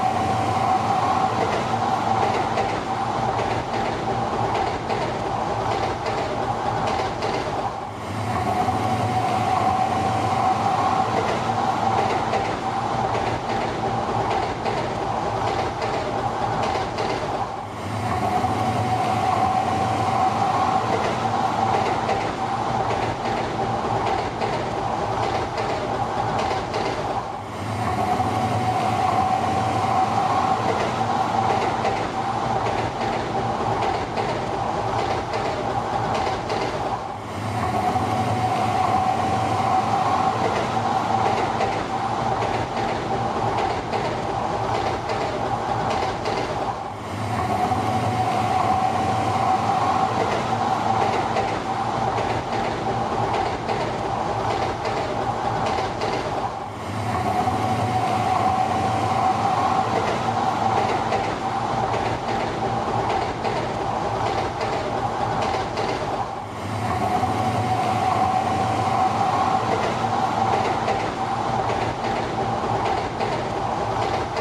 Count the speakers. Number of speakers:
0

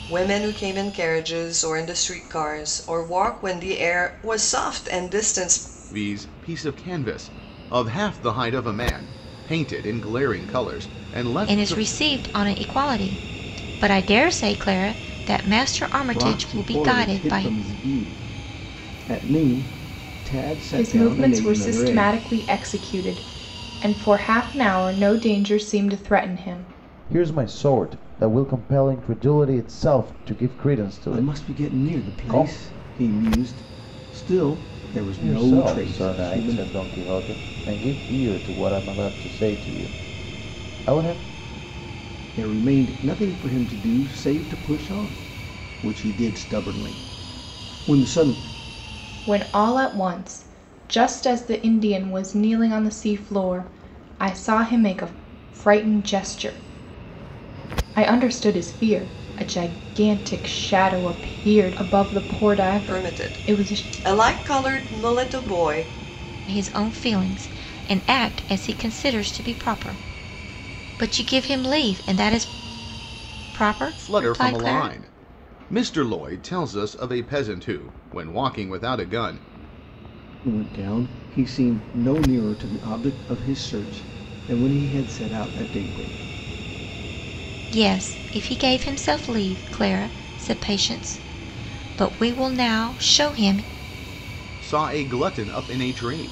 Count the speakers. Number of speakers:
6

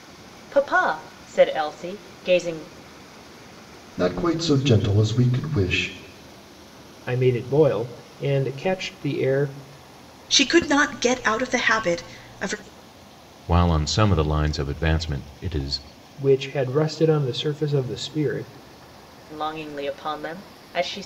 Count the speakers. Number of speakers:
5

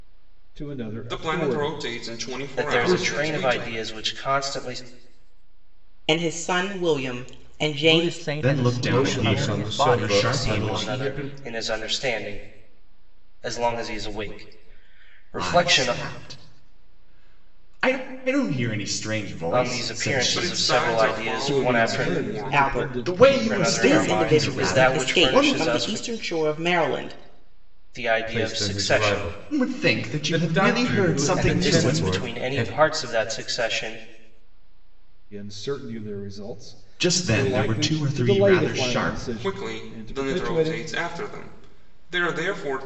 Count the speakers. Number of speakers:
7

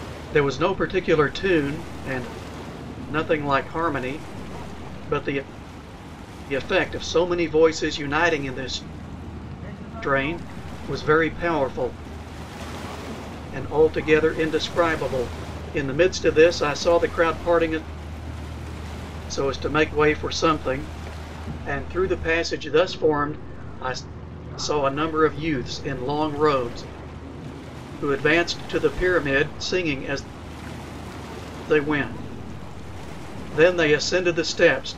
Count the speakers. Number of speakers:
1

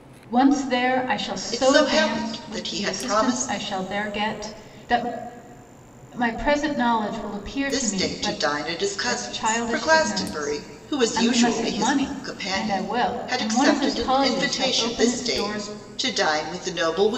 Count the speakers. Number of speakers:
2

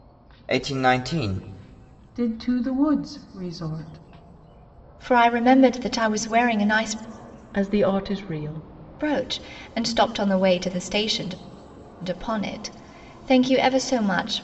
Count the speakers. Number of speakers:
4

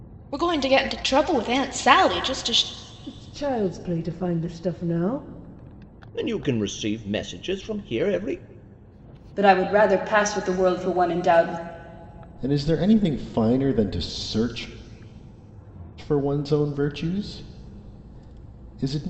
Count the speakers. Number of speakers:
5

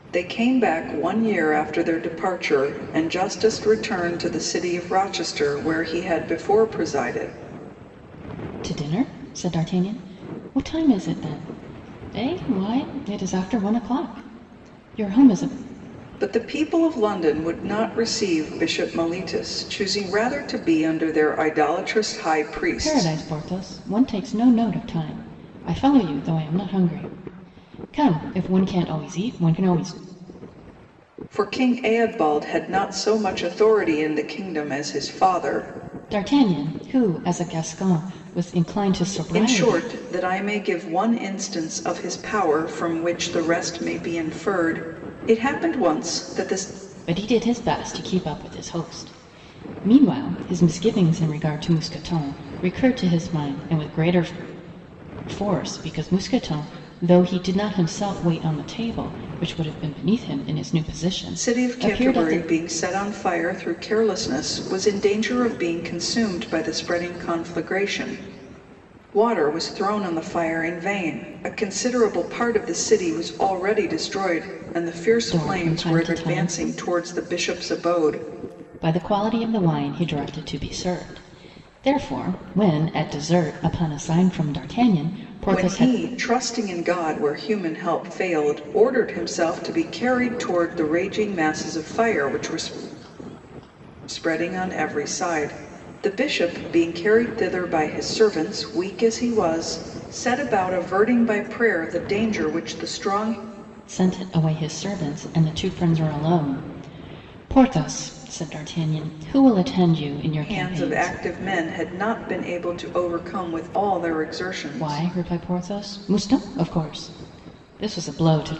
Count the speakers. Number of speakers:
2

